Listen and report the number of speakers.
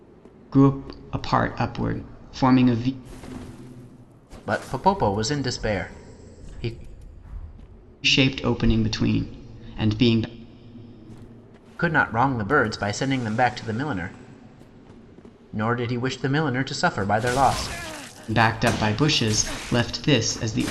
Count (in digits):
2